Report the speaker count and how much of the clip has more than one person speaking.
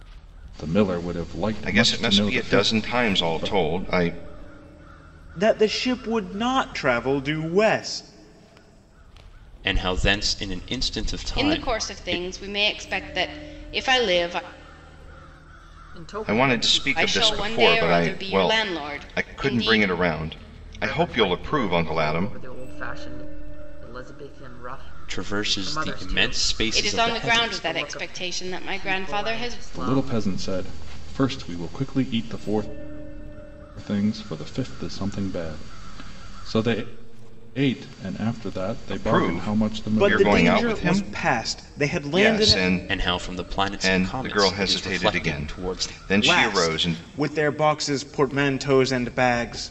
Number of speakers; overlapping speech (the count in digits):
6, about 40%